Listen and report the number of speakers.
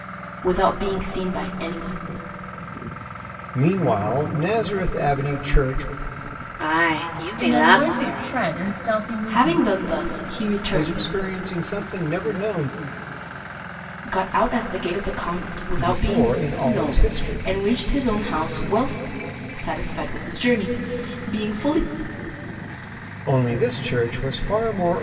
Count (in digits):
4